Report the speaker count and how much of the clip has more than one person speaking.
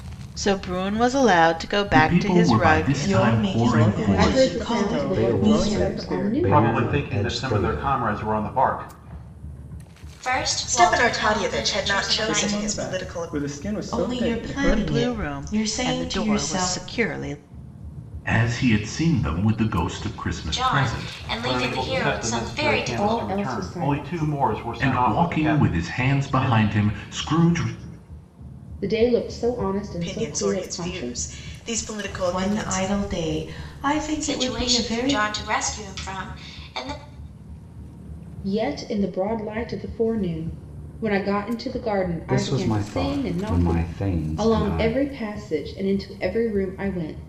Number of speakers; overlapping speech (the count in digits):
9, about 48%